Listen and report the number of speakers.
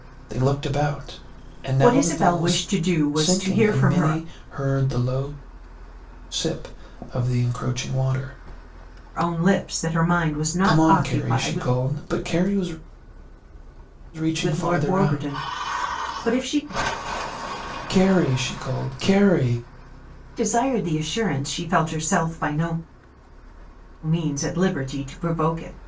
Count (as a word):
two